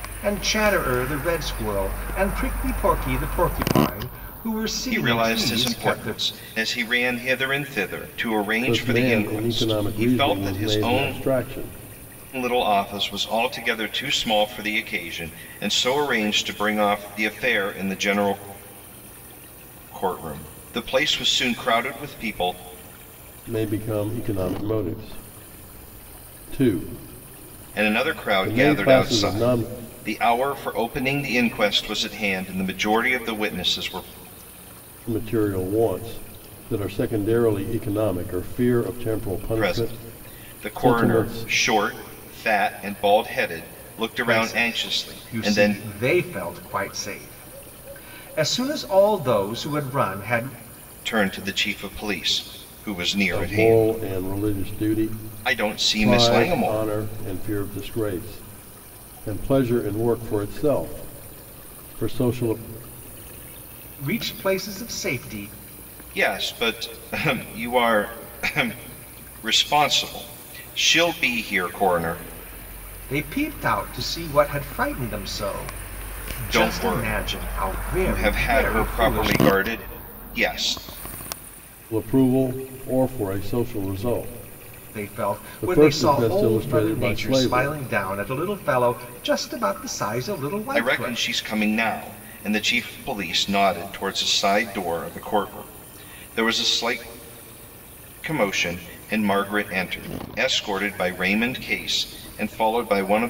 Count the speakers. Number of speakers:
three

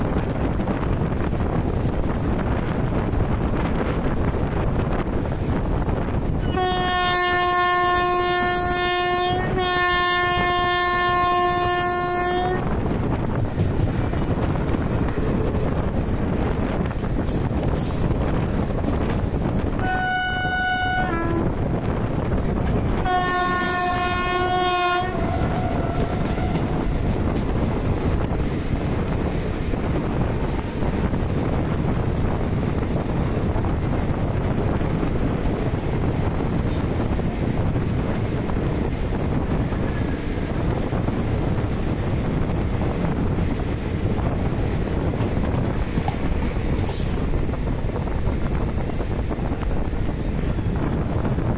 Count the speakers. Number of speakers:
zero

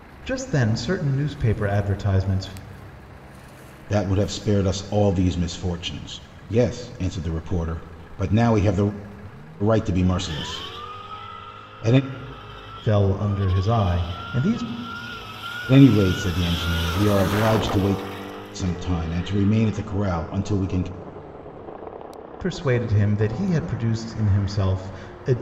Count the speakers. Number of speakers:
two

